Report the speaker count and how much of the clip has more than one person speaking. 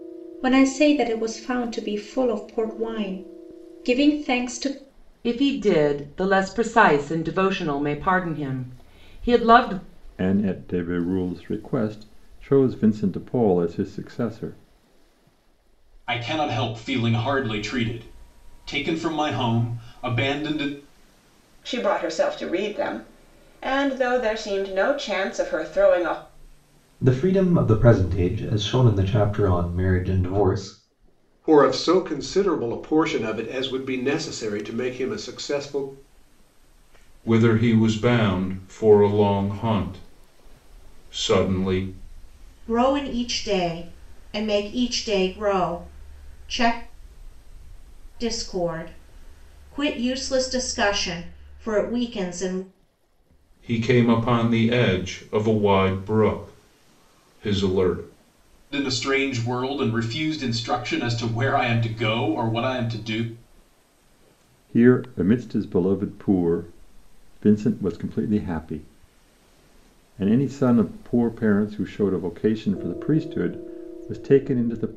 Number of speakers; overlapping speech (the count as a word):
nine, no overlap